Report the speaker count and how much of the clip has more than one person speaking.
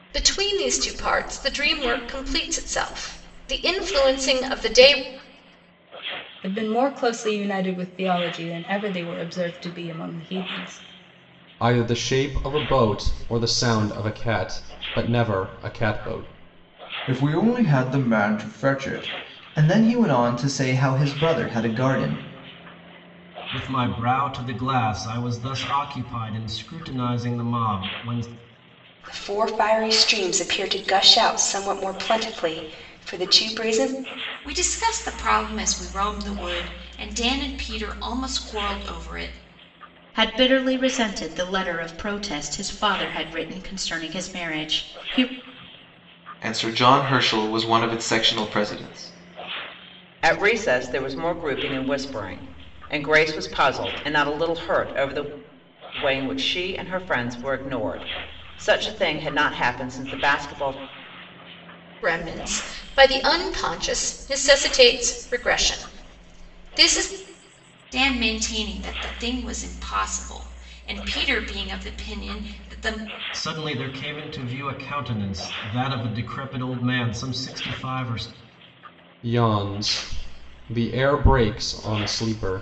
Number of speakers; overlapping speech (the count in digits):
10, no overlap